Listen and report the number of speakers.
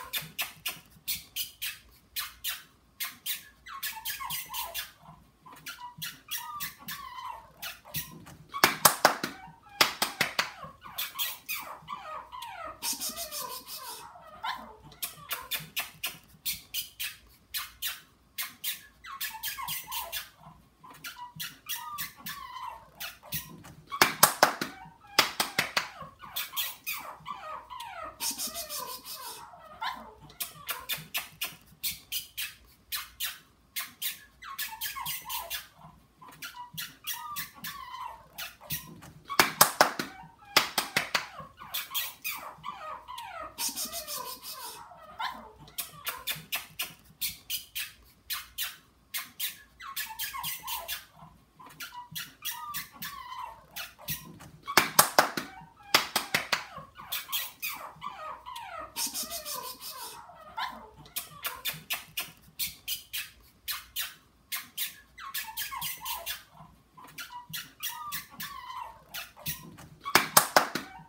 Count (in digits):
0